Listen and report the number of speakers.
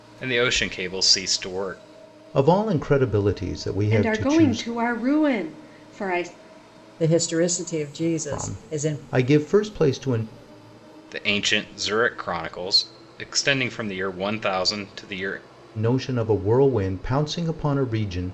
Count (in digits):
4